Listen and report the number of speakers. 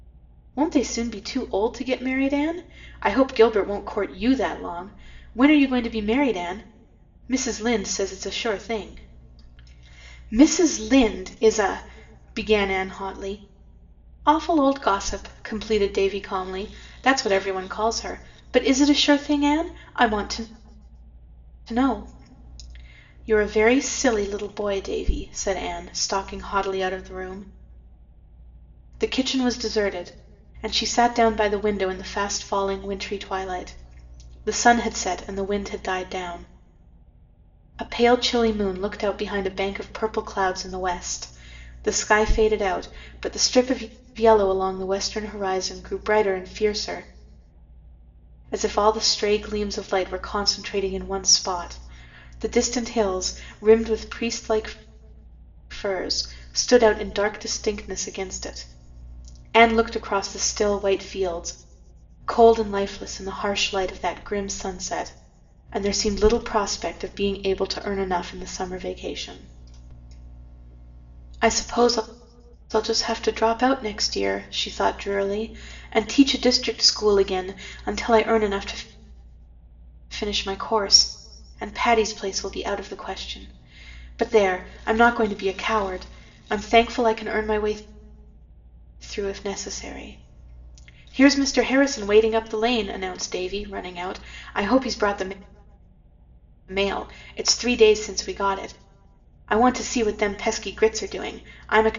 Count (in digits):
1